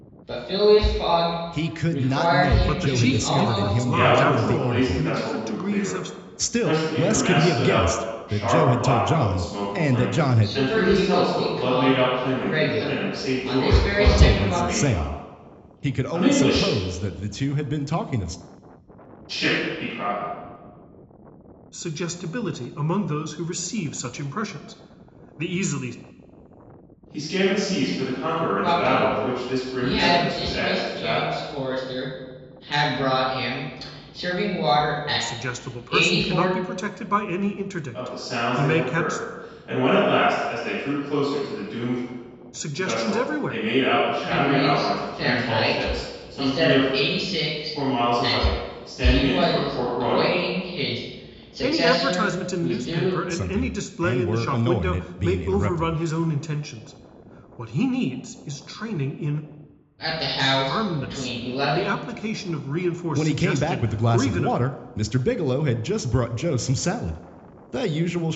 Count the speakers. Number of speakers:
4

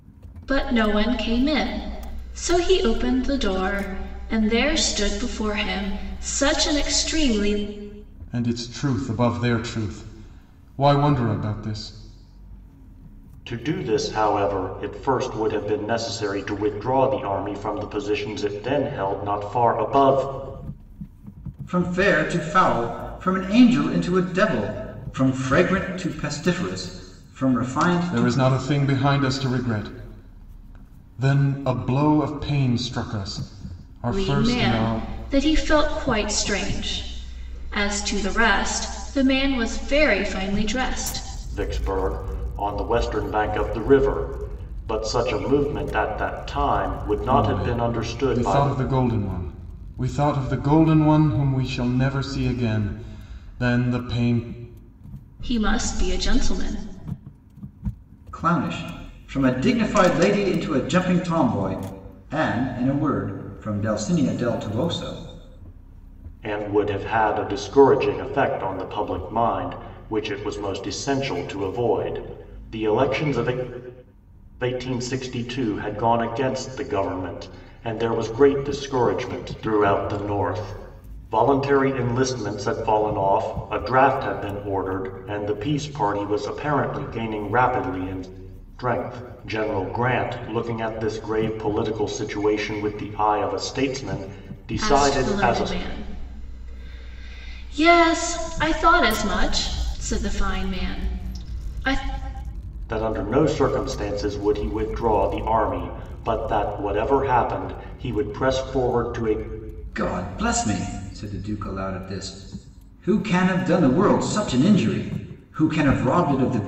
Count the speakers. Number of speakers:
4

